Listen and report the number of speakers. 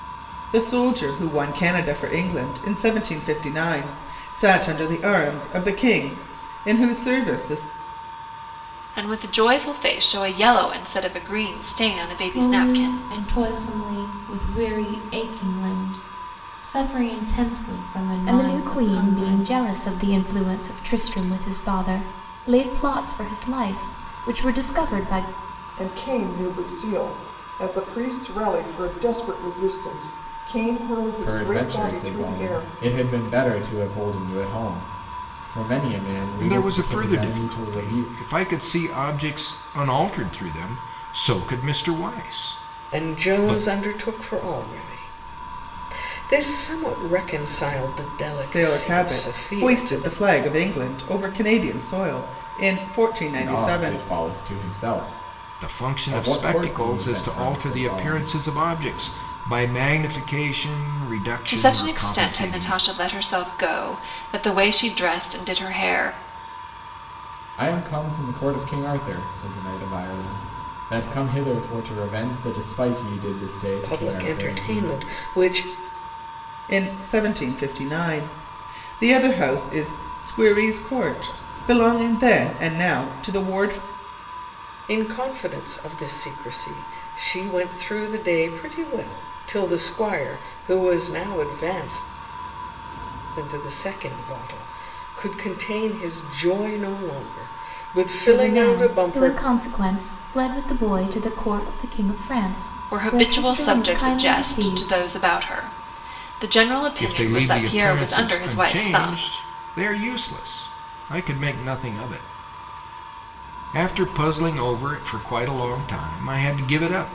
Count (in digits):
8